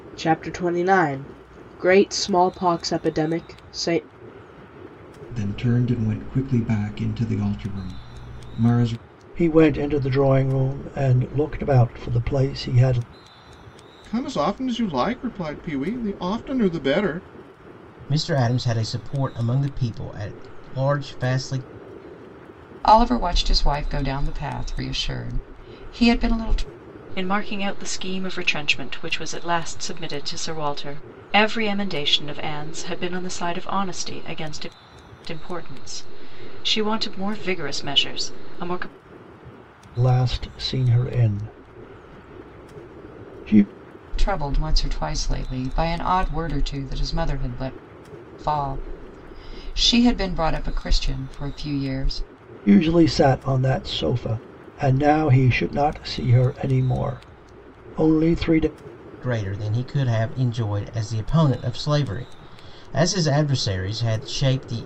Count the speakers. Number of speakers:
7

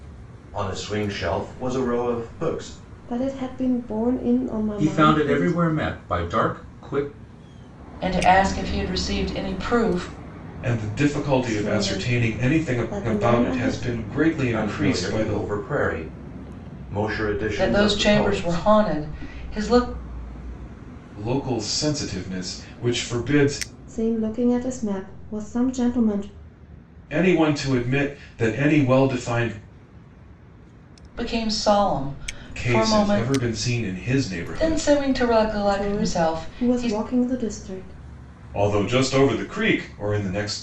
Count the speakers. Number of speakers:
5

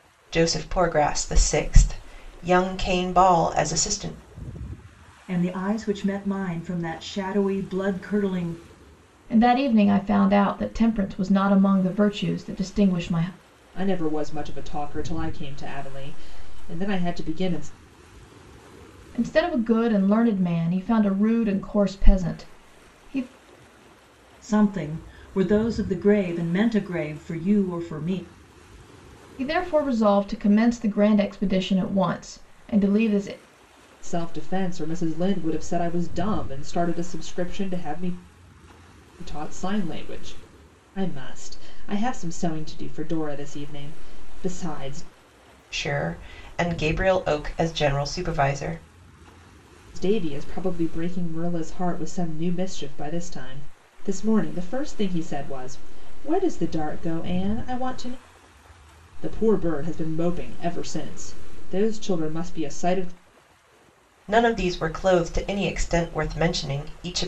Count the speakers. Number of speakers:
4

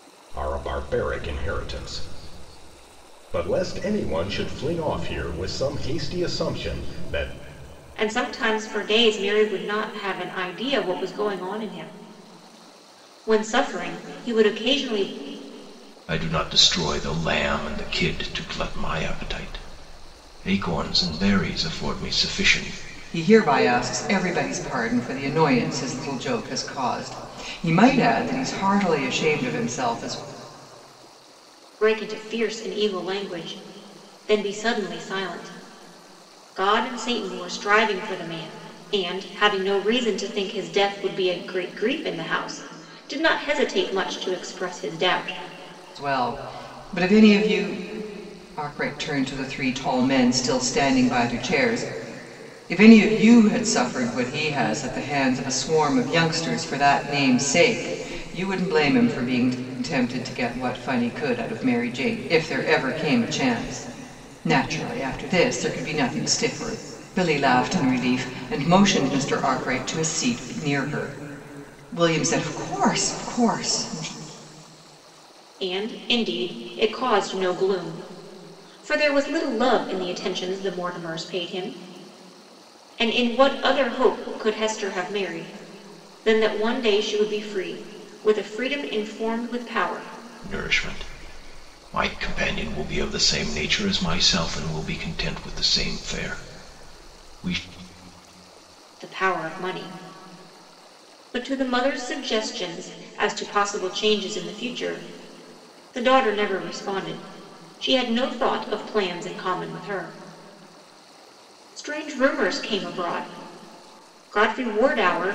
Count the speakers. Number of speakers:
4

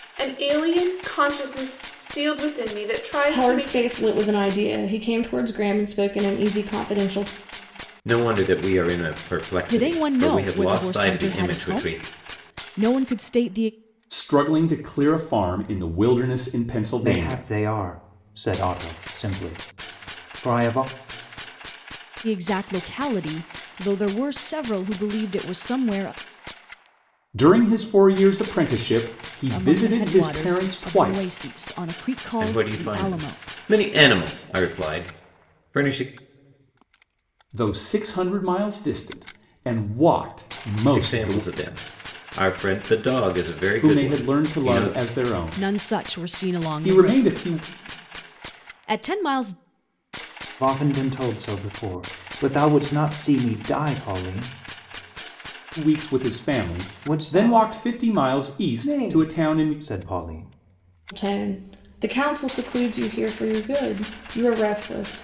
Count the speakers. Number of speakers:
6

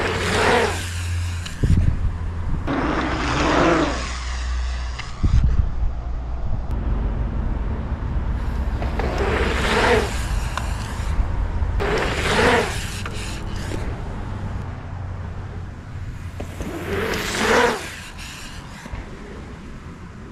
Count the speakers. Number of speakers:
0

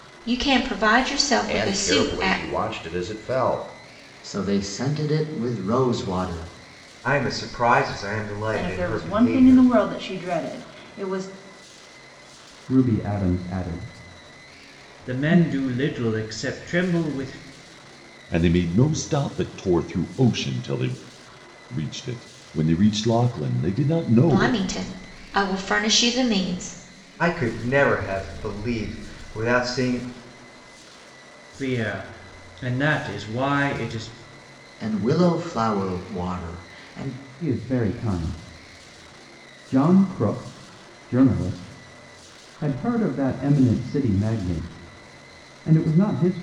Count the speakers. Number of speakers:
8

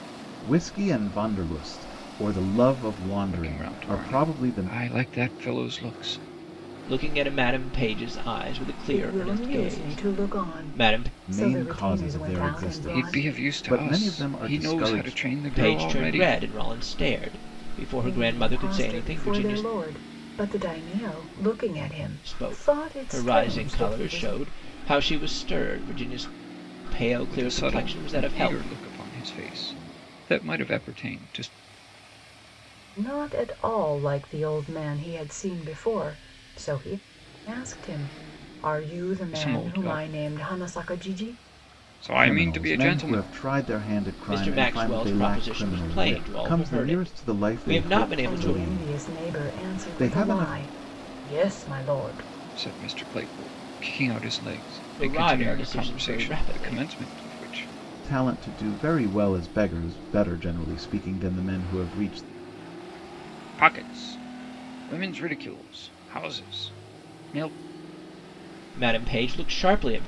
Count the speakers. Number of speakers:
4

